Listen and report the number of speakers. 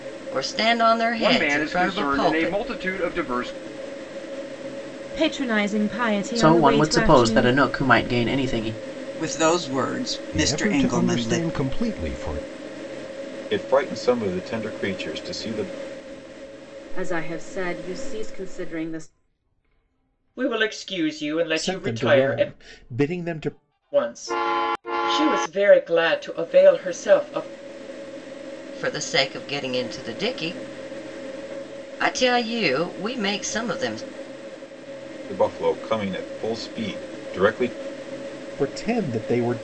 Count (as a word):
ten